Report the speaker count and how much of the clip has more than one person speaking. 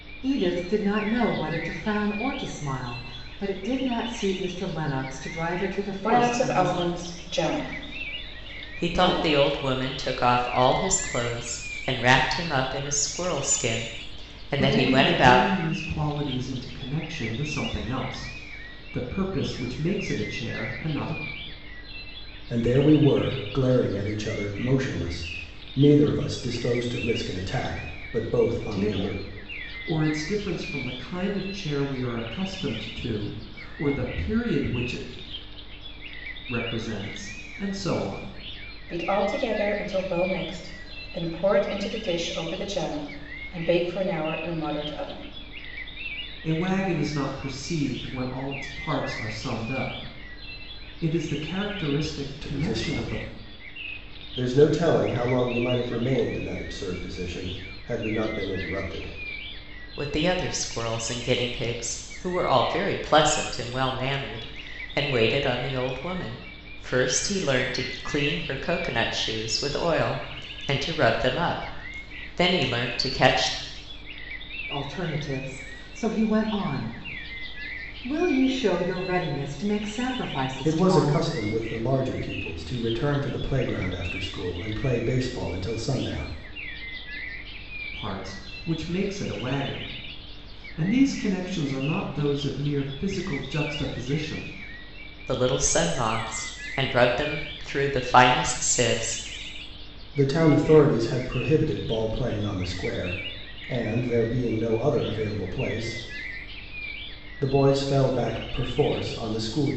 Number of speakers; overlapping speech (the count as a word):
five, about 4%